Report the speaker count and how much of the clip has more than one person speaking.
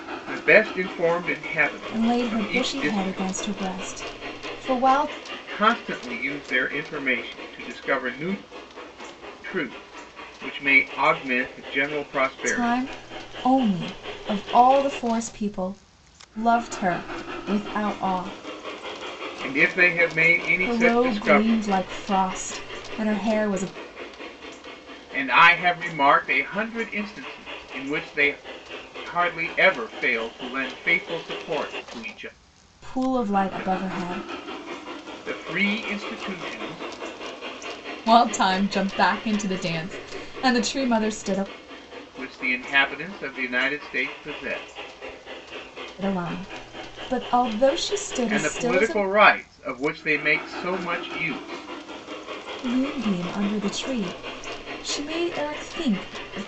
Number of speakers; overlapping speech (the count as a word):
two, about 8%